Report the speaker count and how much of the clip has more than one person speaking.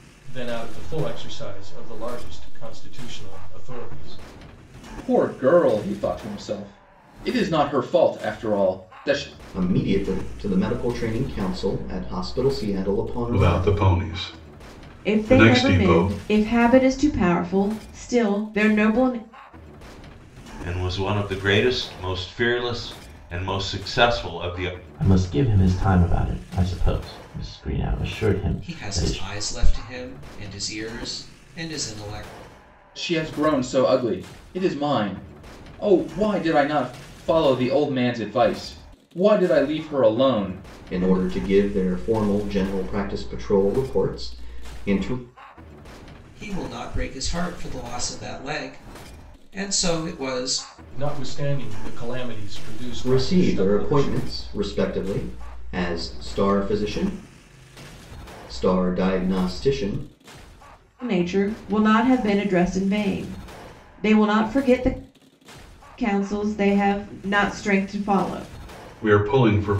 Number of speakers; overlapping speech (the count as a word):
eight, about 6%